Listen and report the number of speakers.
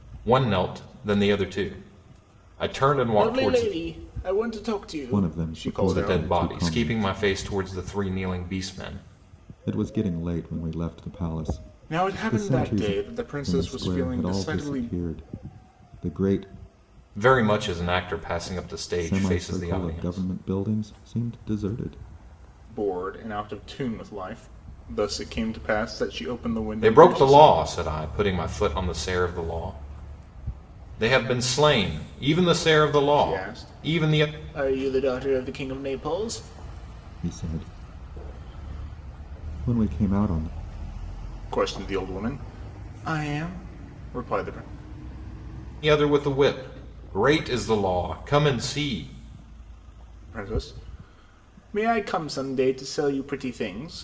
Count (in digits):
3